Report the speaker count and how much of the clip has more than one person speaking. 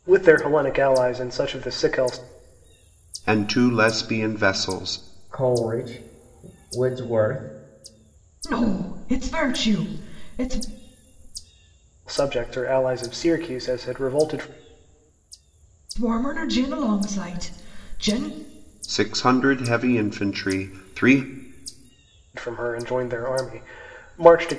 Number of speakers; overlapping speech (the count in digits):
4, no overlap